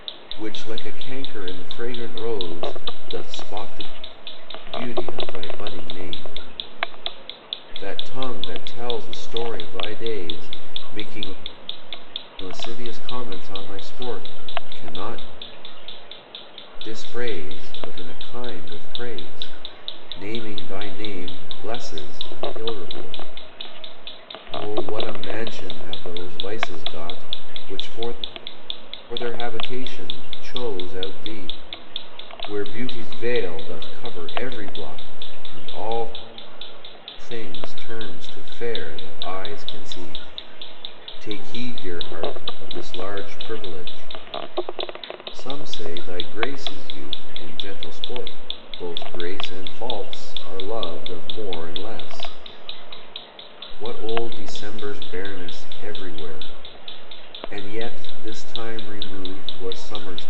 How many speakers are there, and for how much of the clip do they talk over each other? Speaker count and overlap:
1, no overlap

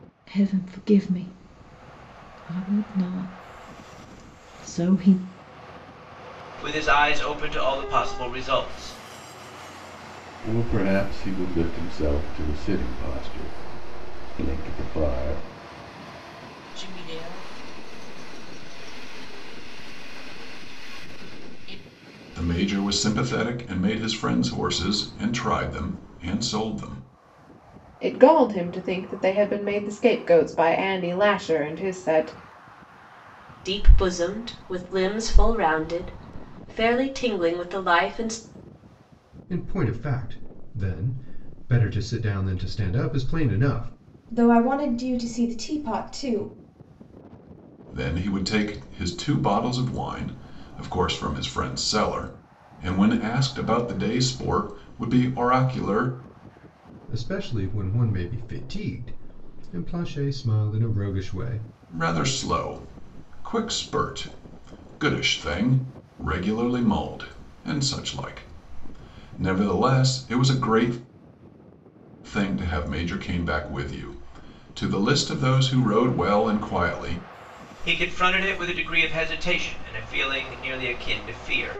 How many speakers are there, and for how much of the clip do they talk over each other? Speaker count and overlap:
9, no overlap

